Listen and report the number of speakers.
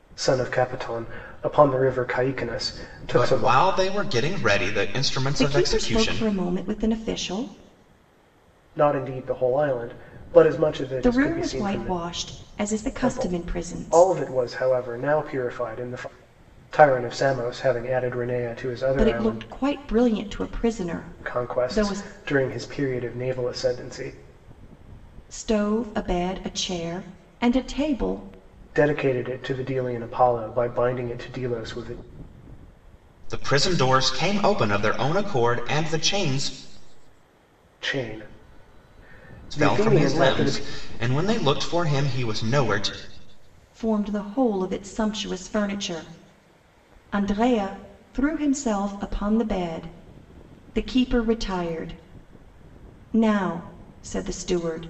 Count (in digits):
3